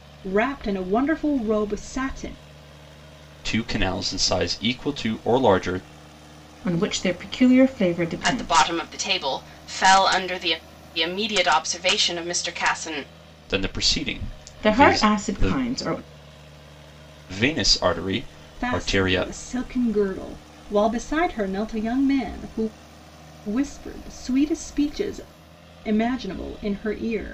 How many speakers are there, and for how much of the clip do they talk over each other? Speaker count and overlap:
4, about 8%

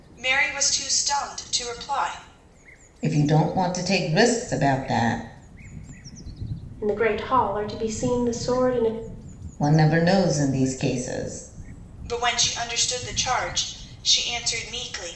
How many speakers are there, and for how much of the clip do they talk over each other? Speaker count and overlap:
3, no overlap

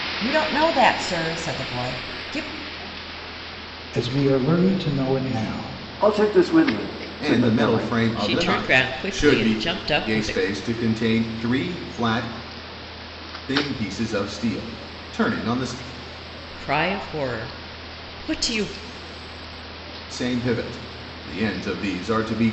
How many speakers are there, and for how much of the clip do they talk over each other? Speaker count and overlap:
5, about 12%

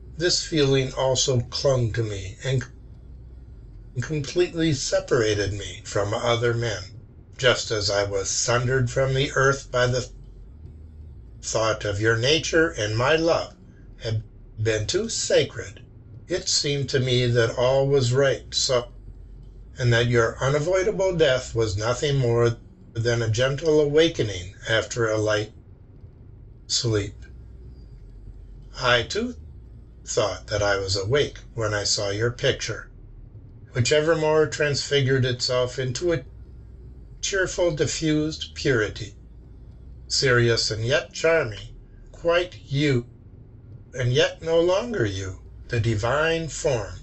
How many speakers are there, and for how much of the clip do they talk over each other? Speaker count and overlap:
1, no overlap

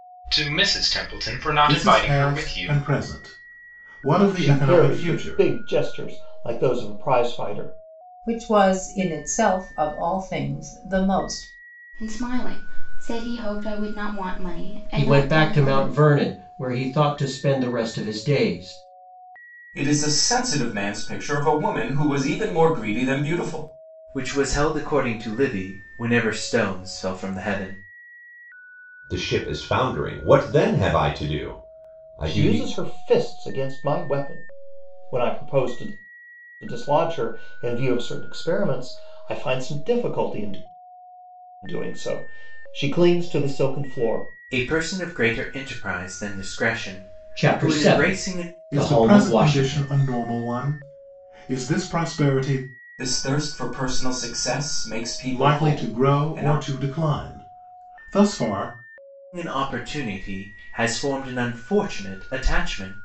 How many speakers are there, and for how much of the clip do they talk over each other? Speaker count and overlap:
9, about 12%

